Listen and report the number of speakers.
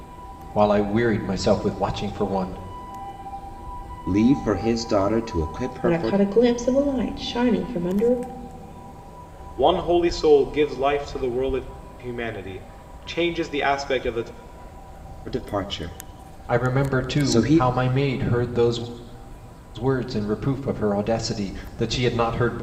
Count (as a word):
four